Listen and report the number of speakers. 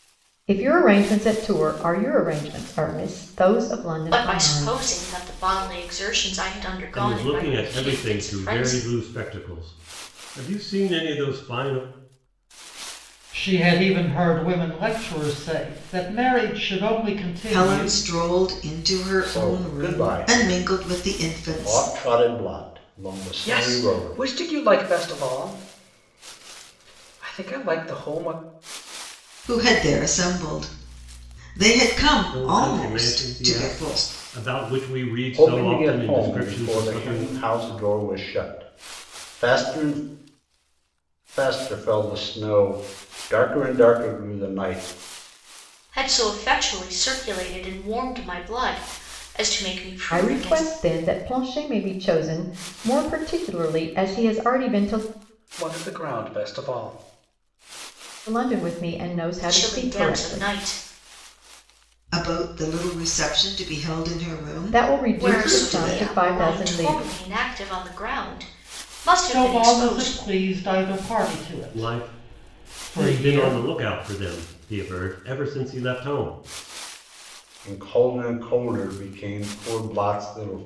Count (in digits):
7